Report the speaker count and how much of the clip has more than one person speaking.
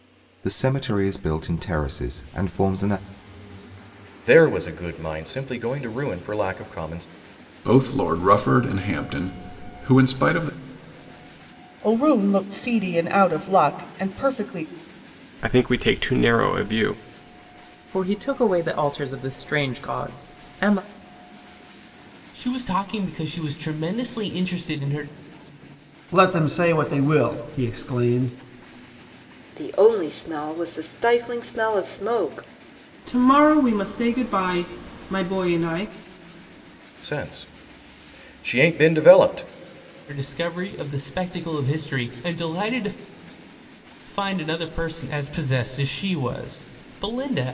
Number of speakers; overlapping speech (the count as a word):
ten, no overlap